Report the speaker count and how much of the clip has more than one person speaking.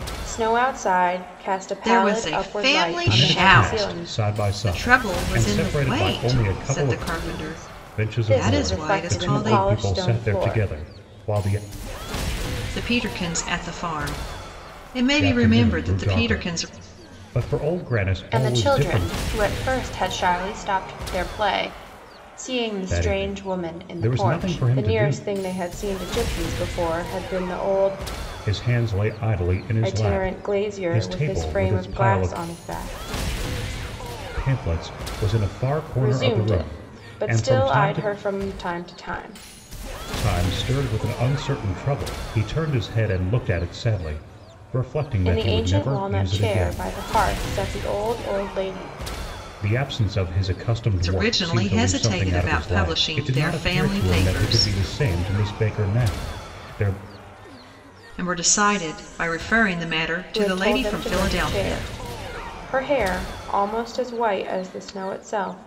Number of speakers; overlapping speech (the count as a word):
three, about 38%